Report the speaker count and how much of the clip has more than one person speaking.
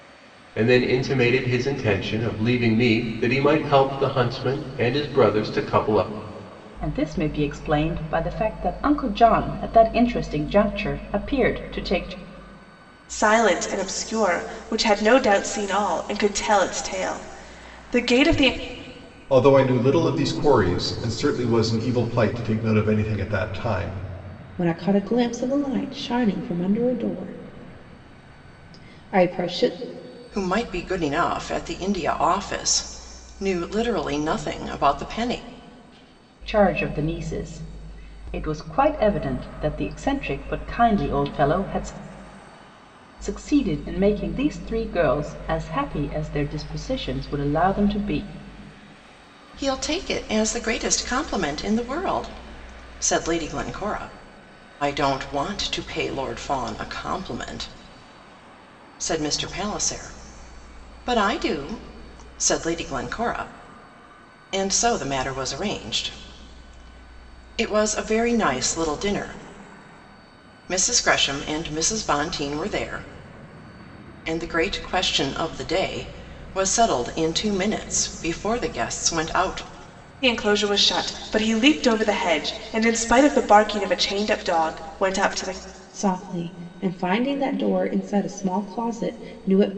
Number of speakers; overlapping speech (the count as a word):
six, no overlap